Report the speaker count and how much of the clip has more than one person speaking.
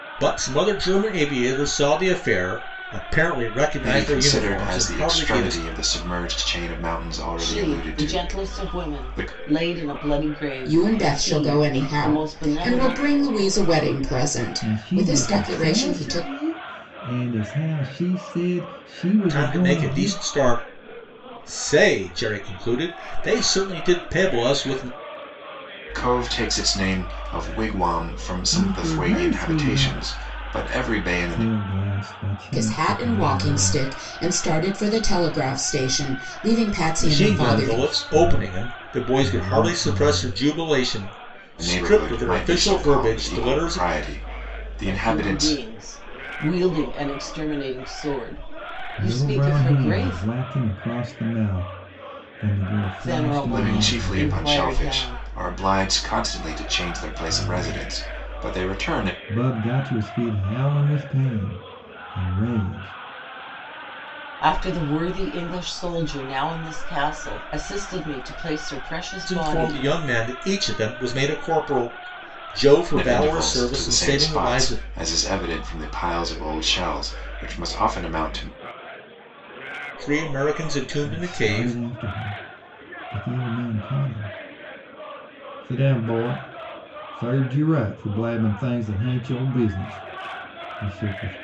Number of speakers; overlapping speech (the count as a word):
five, about 32%